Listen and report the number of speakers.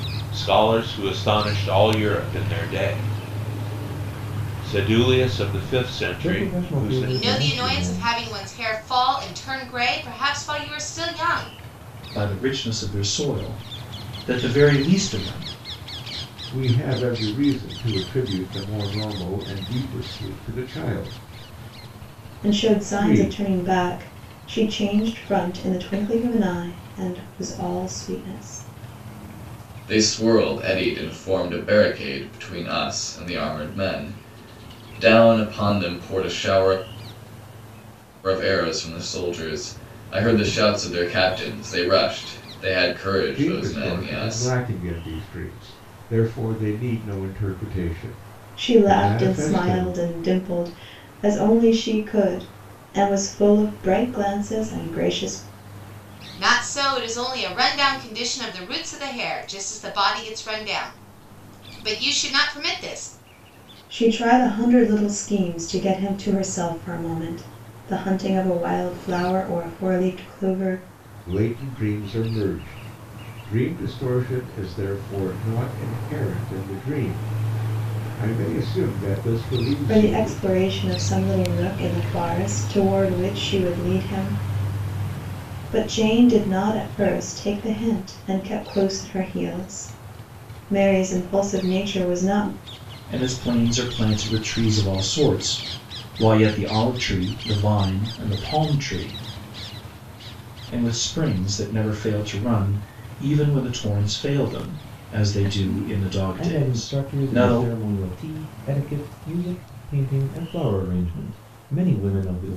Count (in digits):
7